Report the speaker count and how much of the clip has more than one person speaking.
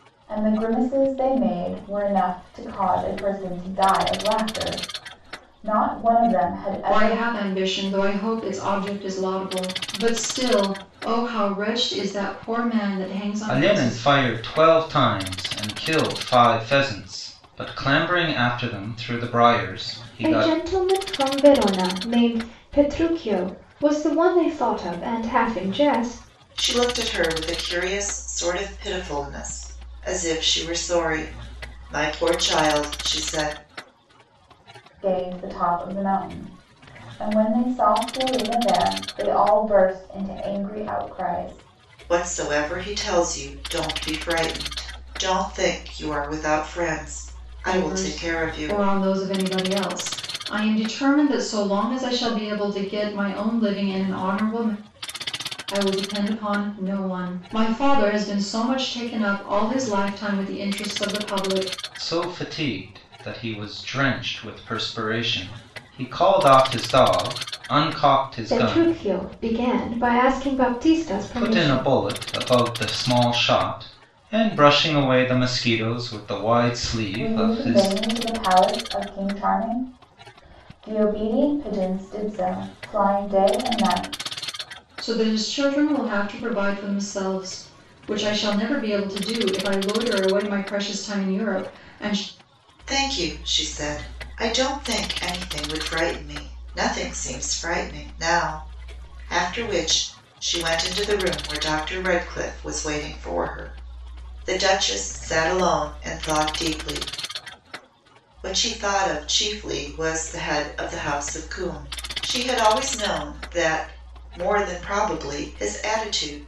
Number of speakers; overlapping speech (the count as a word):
five, about 4%